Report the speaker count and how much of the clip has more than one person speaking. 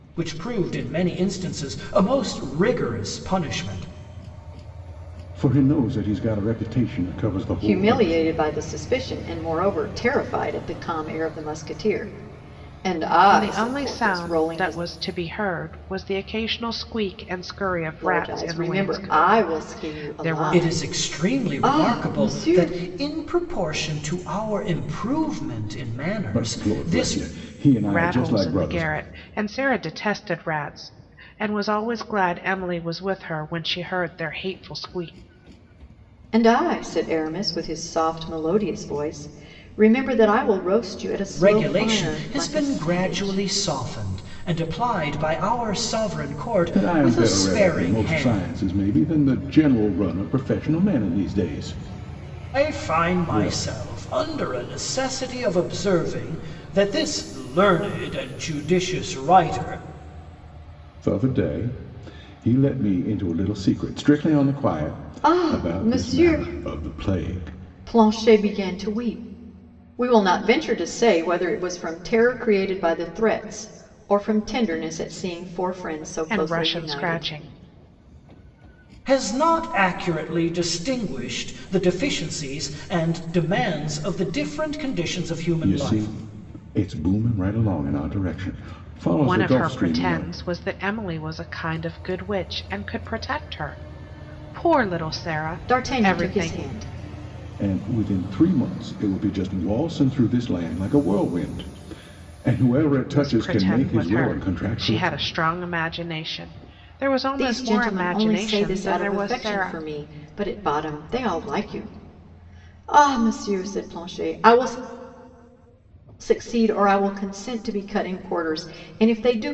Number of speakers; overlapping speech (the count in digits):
4, about 21%